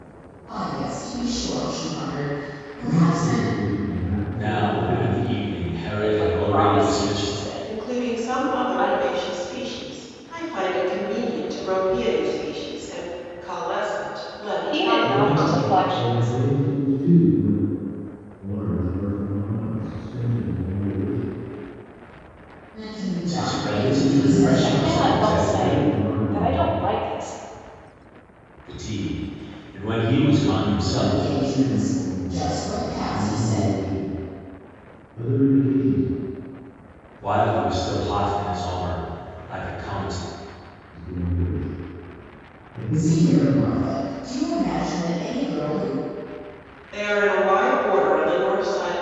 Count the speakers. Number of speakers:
5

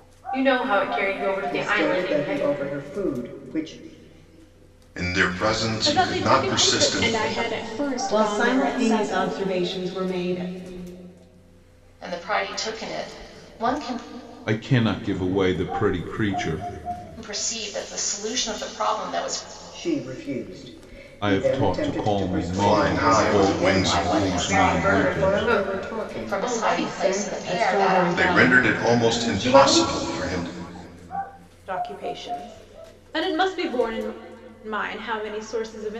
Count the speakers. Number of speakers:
8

